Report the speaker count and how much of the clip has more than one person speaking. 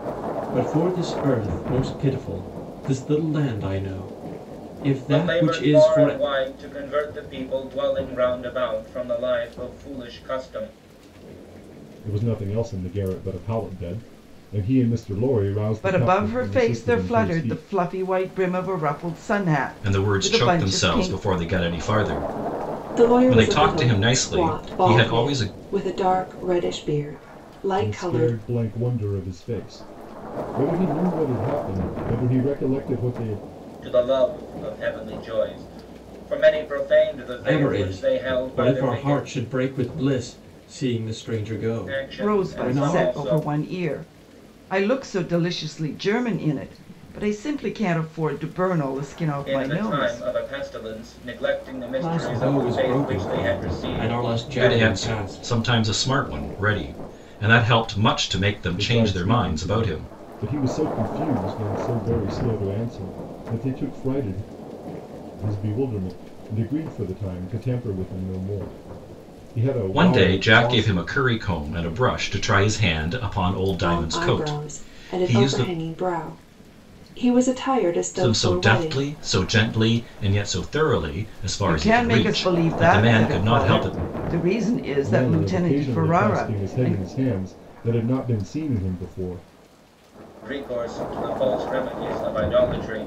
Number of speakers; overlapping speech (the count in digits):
6, about 27%